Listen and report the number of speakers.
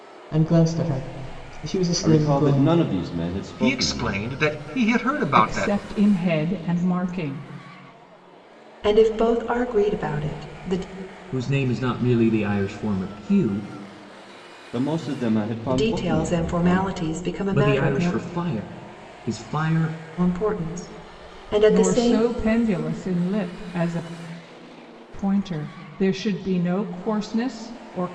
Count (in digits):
6